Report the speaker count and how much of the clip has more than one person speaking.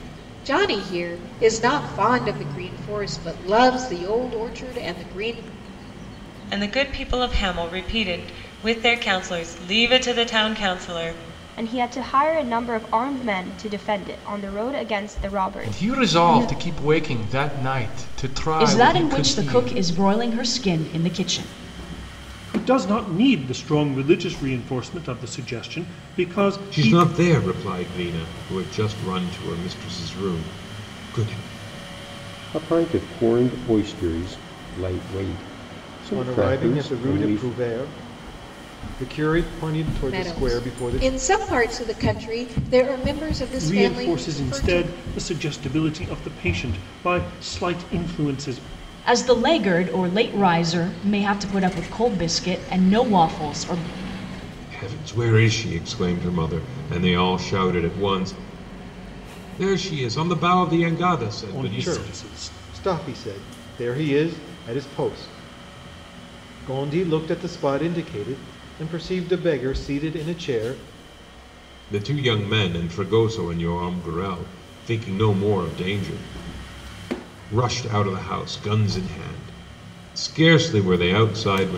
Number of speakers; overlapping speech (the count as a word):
nine, about 9%